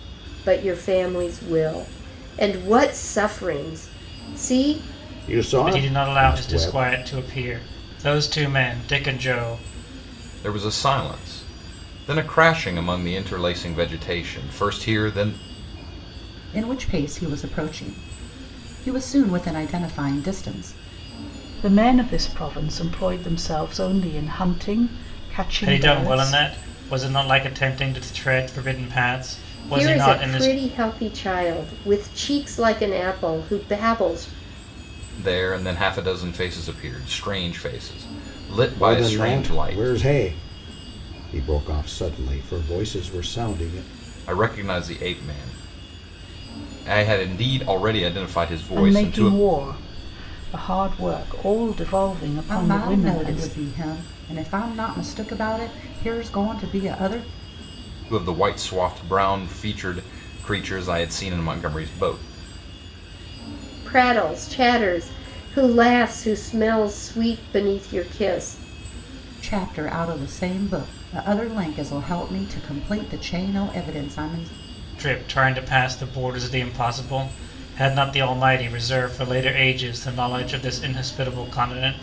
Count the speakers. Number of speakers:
6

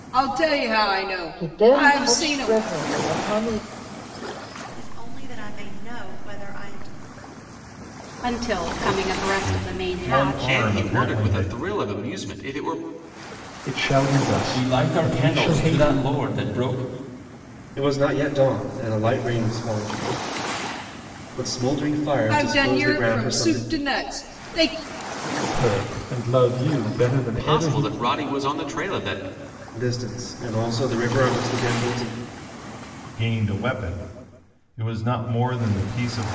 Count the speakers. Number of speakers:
9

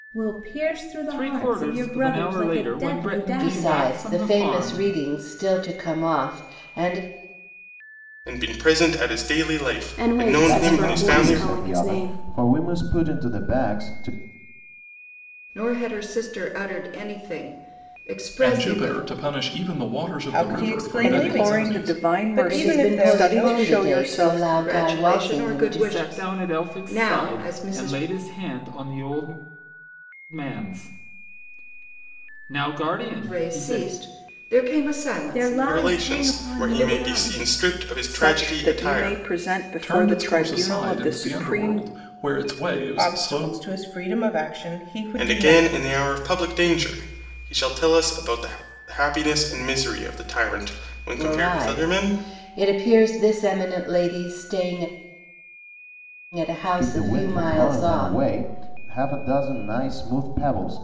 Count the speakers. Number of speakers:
10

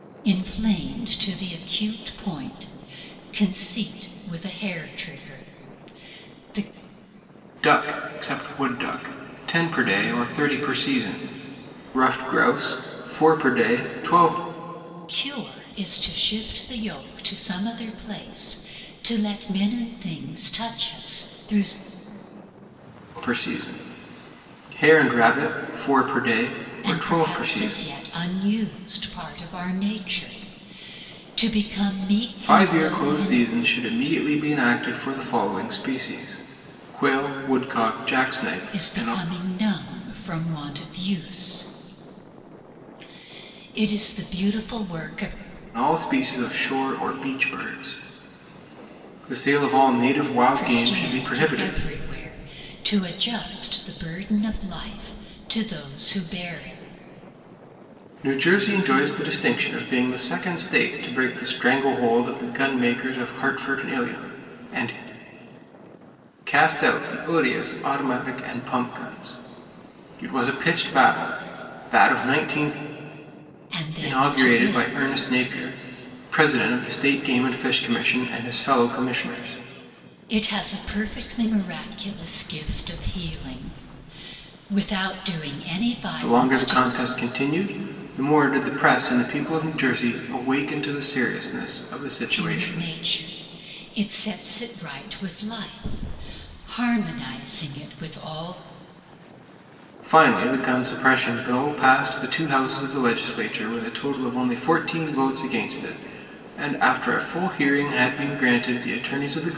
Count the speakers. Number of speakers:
2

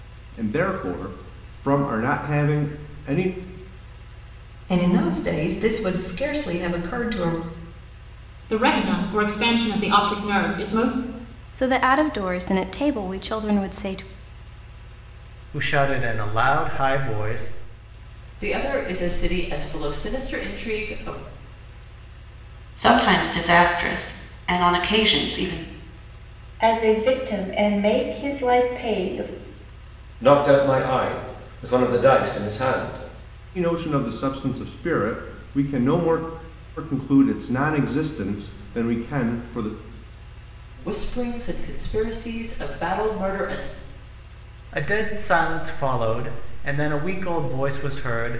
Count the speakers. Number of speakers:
9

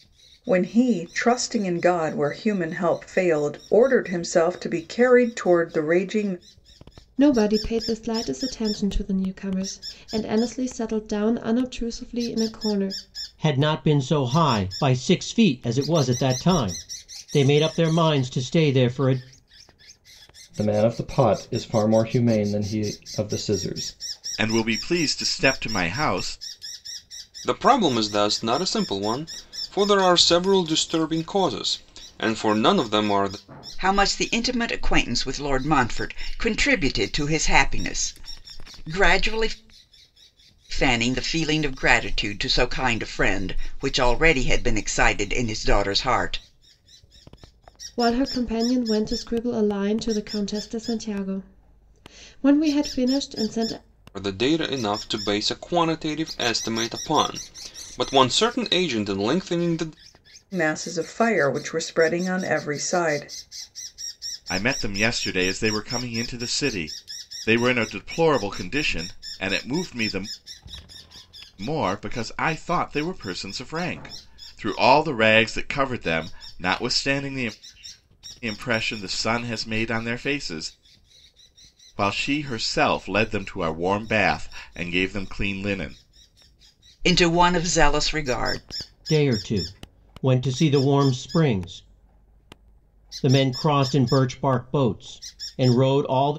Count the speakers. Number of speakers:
7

